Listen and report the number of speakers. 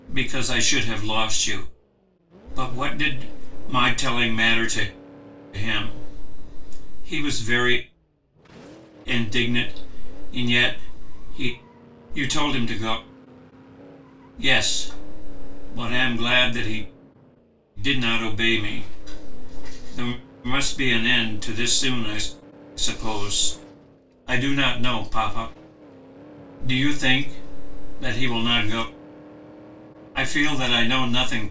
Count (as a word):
one